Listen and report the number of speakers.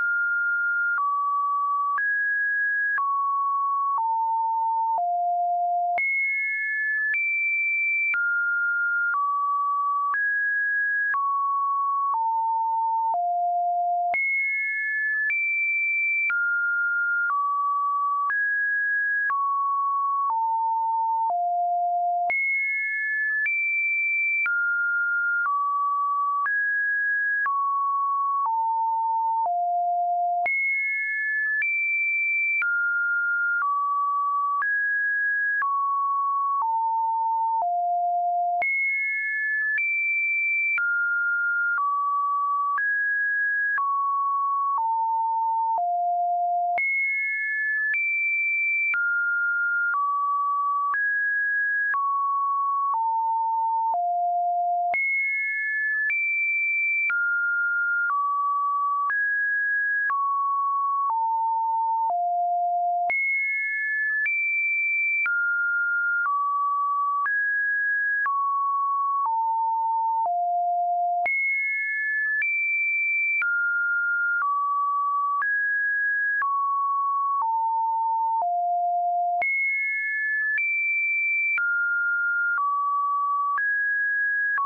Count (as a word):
zero